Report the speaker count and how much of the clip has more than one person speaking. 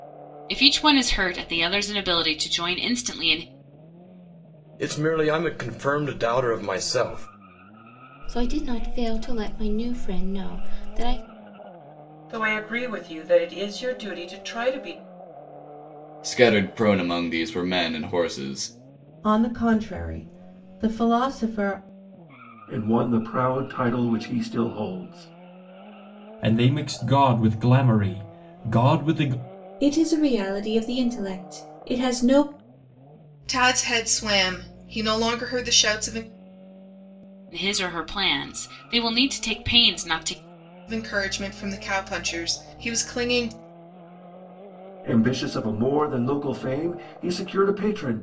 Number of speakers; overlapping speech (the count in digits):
10, no overlap